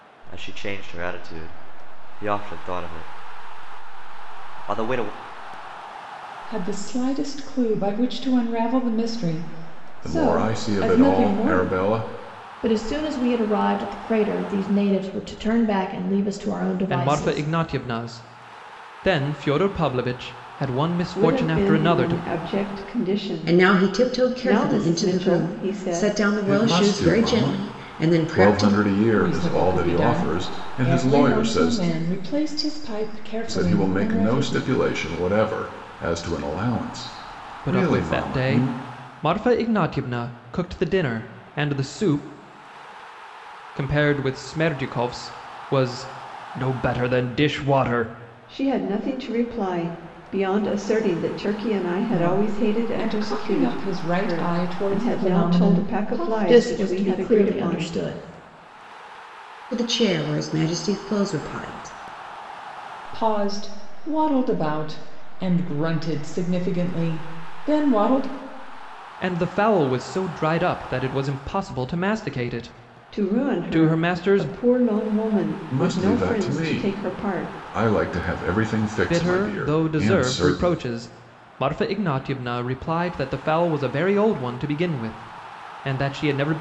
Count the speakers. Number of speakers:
seven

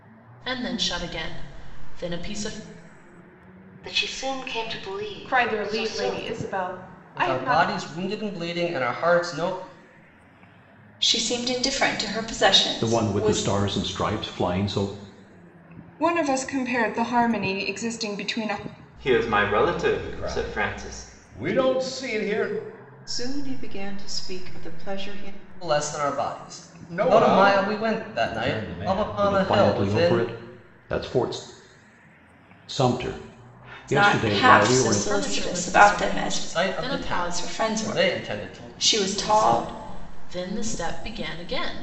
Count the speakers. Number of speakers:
ten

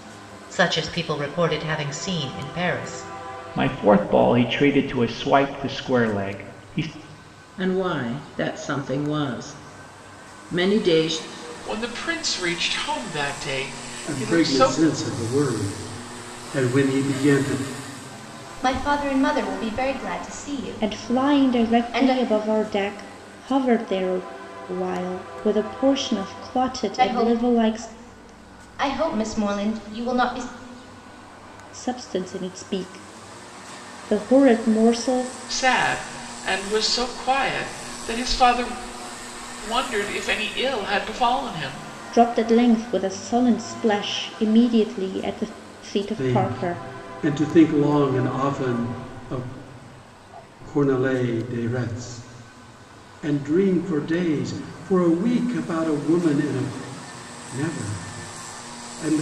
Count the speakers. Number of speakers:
seven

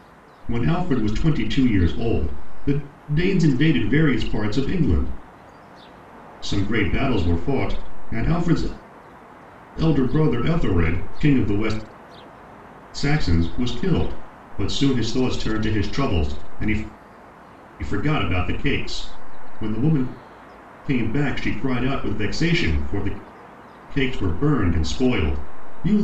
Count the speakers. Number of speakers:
one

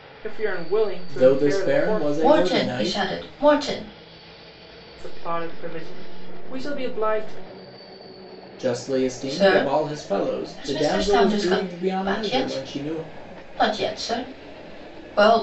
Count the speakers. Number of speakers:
three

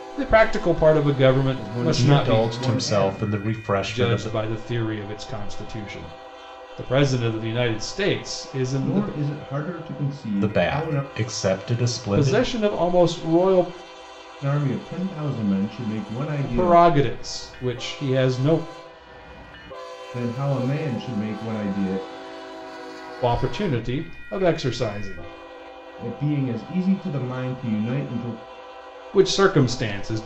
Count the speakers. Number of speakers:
three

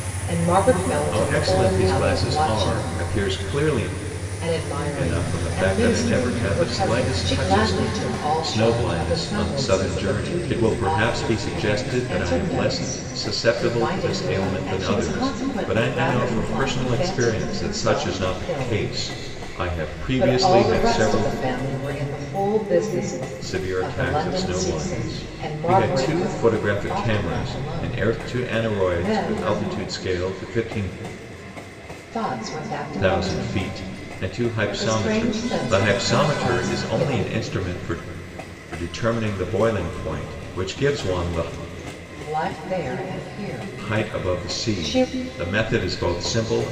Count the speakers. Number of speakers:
two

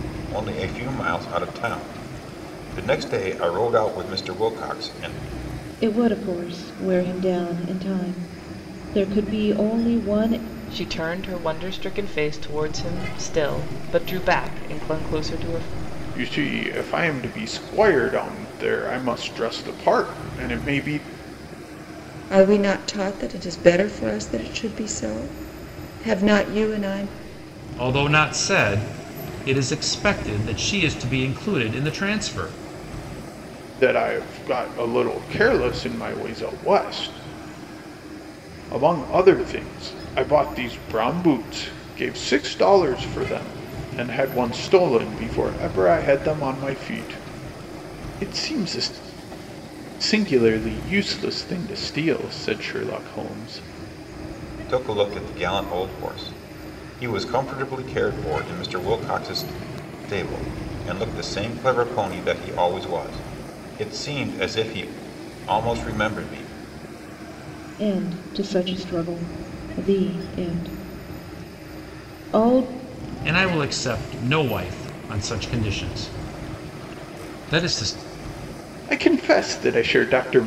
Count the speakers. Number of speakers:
six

